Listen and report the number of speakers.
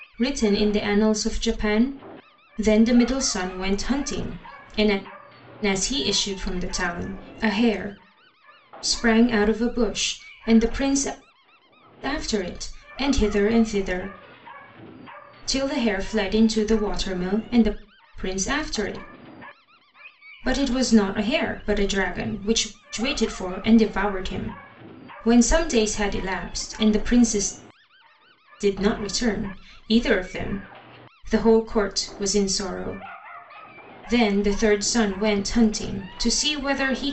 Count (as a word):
one